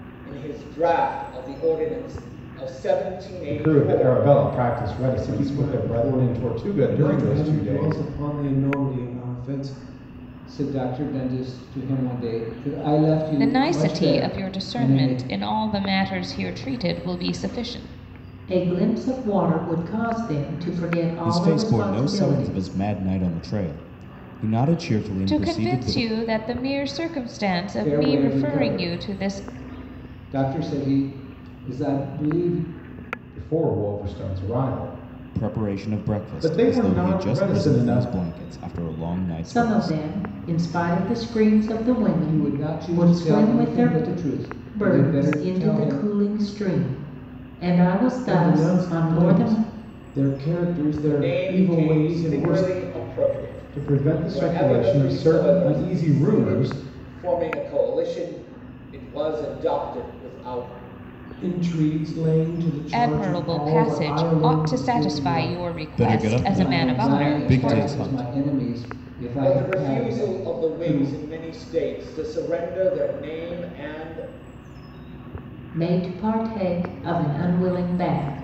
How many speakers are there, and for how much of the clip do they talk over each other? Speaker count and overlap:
7, about 37%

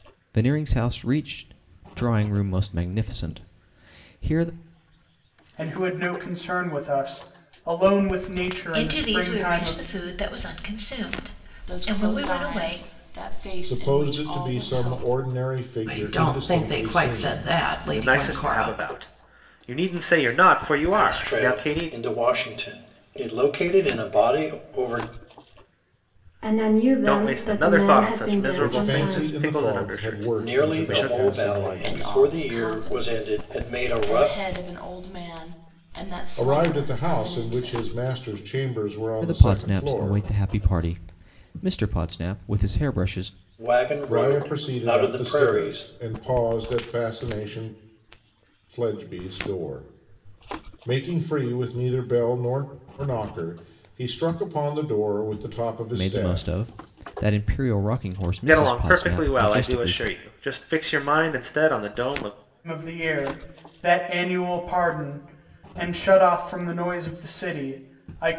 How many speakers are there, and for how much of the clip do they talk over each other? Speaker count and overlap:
9, about 31%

